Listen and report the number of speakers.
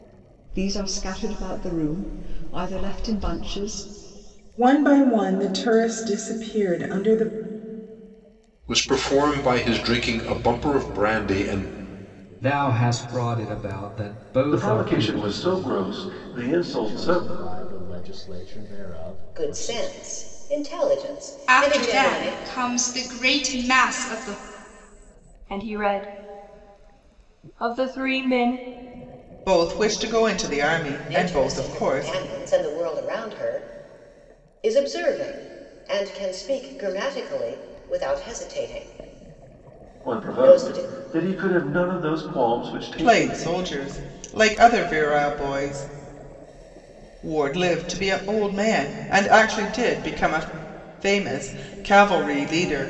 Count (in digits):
10